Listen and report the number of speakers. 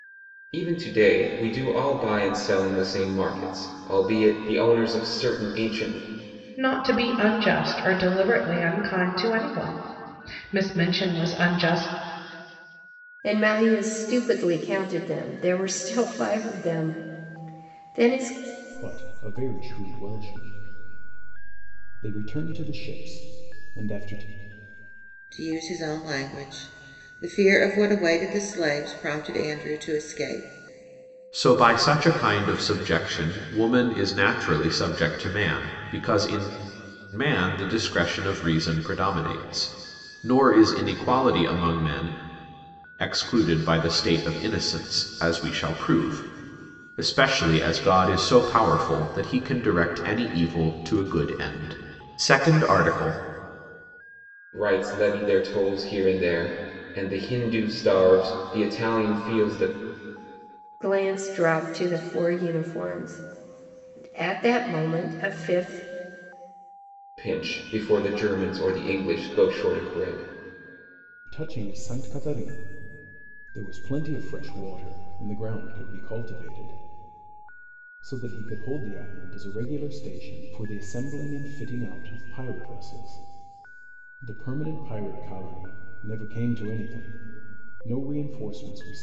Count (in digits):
6